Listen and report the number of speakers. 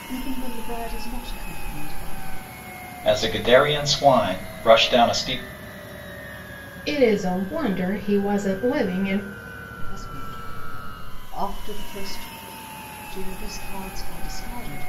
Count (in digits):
3